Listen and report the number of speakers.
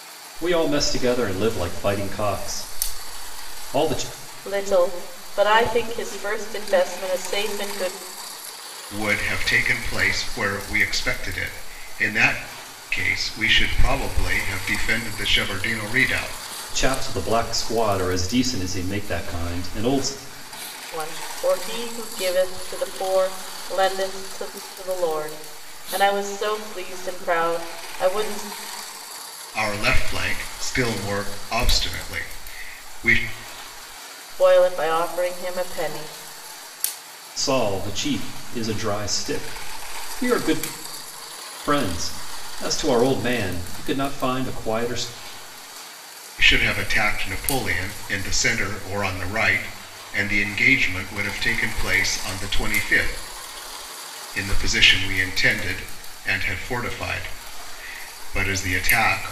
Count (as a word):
three